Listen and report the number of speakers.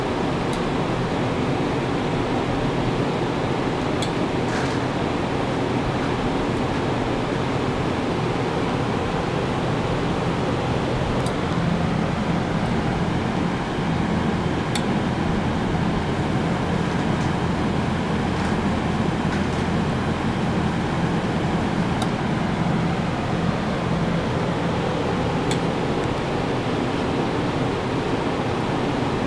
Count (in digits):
0